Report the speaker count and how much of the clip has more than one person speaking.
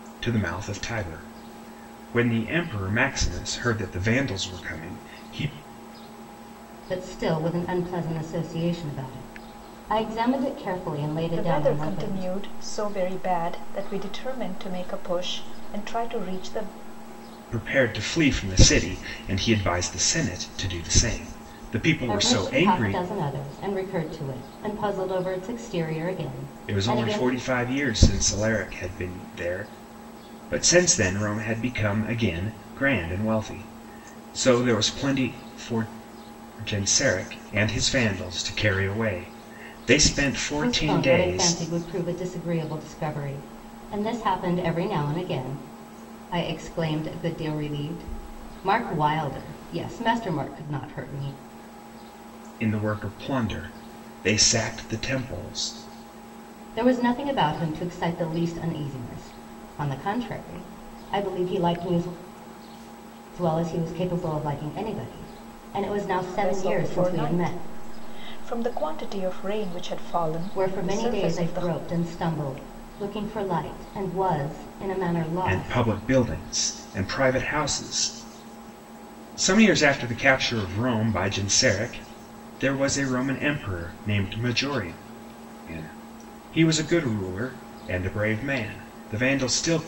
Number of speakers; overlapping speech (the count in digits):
3, about 8%